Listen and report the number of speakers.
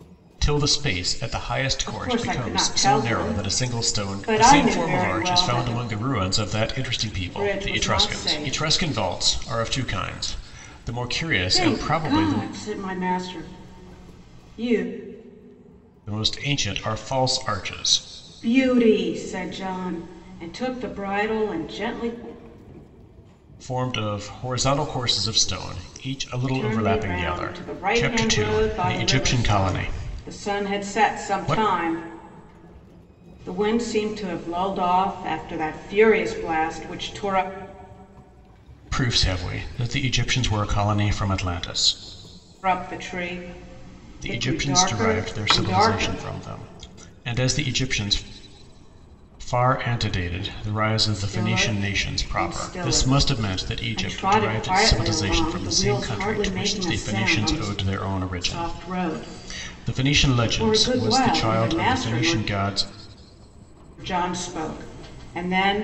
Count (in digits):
2